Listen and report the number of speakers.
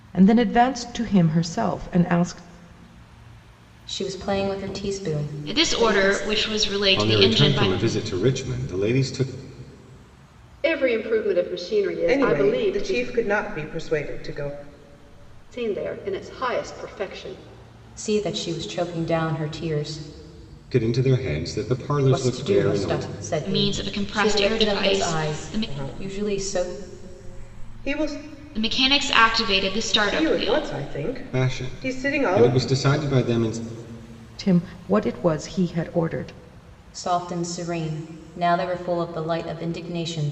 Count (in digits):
6